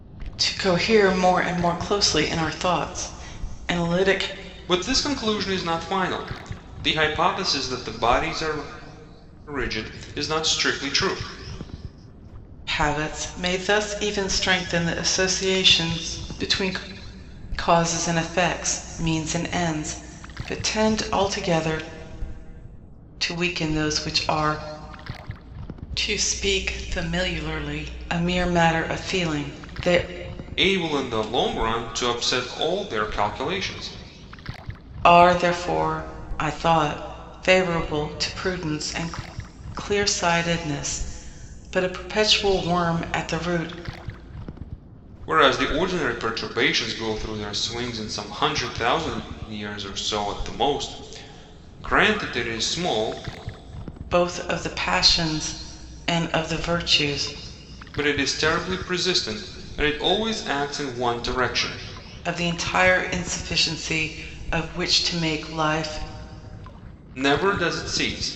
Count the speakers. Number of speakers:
two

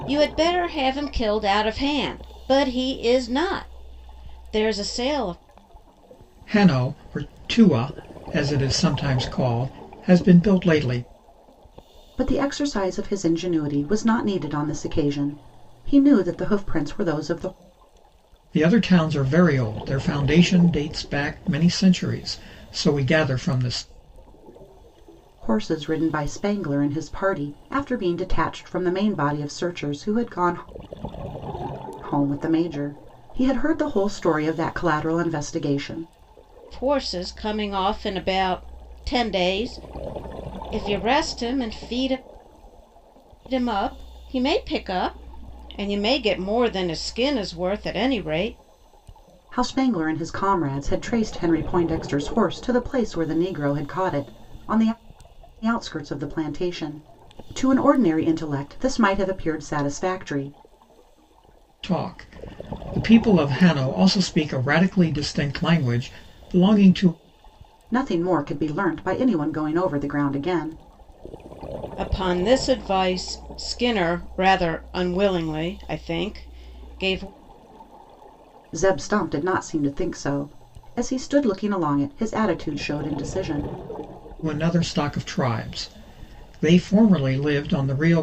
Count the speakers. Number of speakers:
three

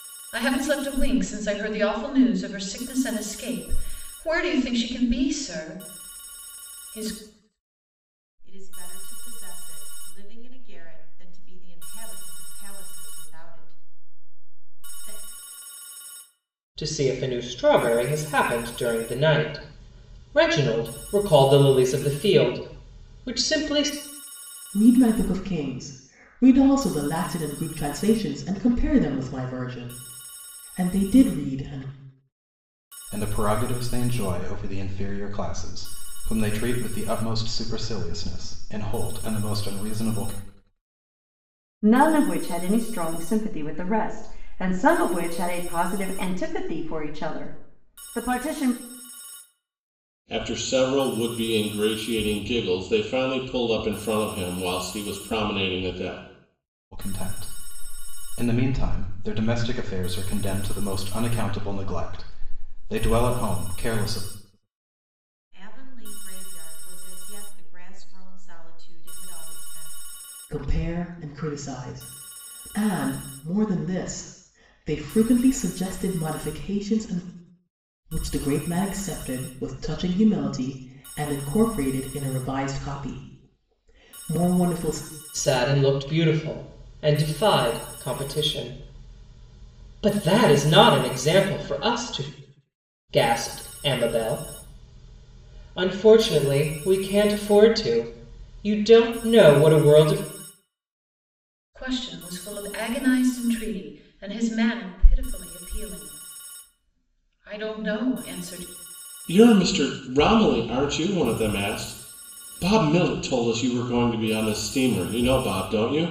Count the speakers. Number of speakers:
seven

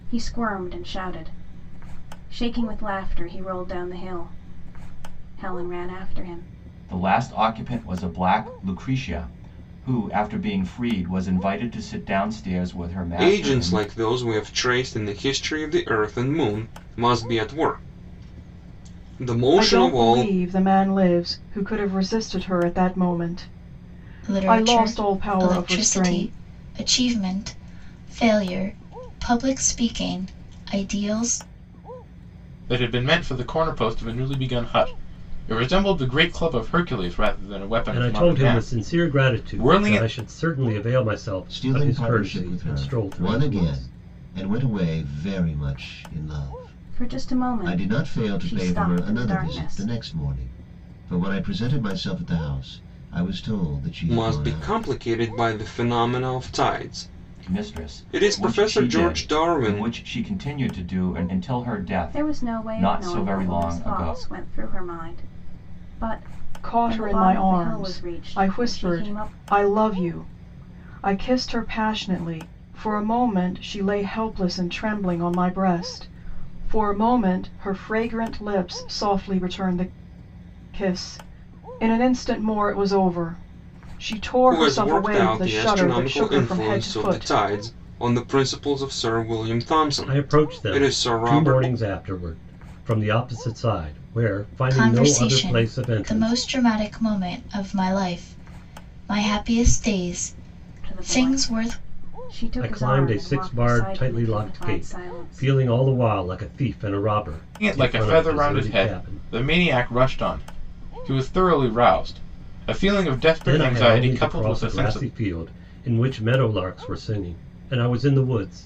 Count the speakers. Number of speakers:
eight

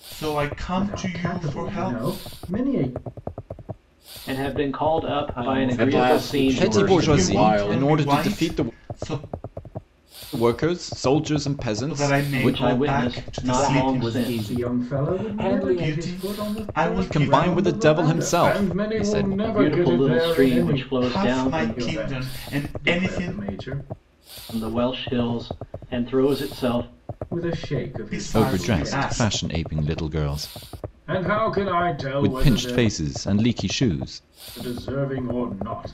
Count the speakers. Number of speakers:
six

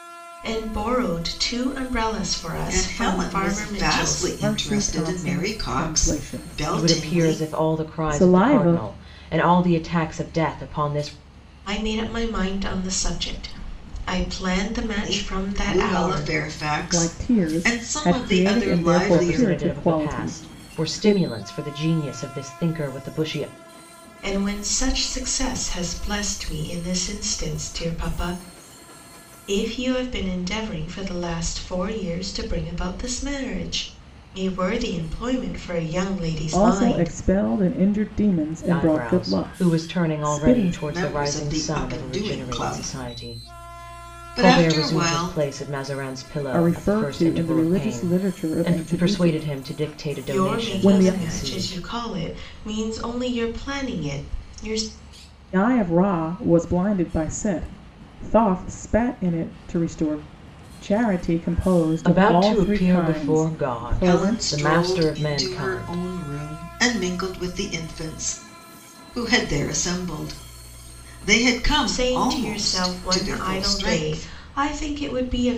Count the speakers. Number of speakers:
four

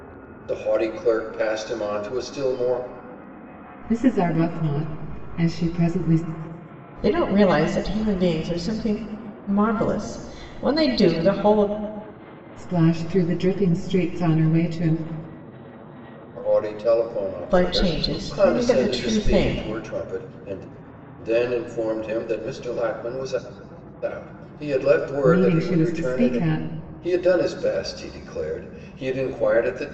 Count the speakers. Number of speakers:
three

